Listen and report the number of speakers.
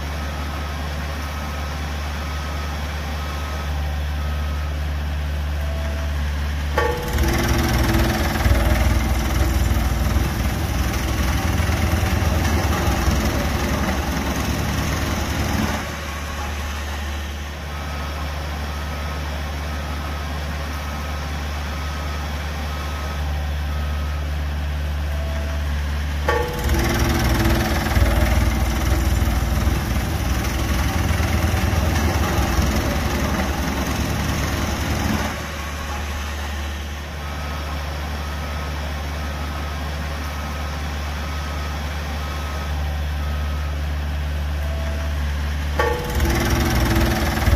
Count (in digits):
0